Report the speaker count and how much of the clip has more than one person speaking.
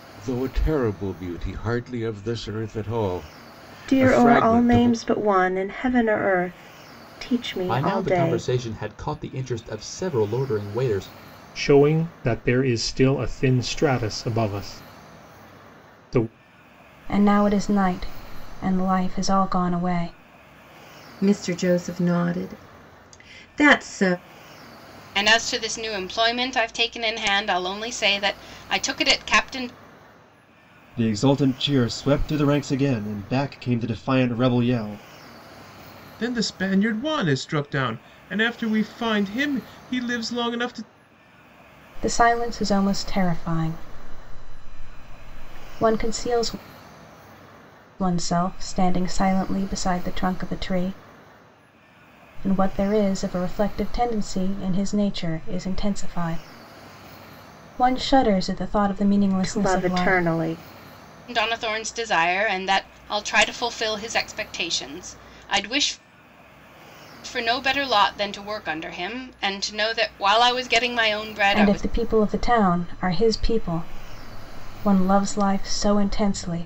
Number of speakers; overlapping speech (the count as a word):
nine, about 4%